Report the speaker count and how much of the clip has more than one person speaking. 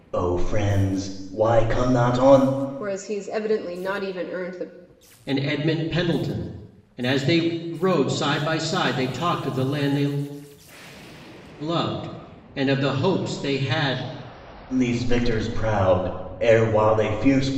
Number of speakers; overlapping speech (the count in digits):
3, no overlap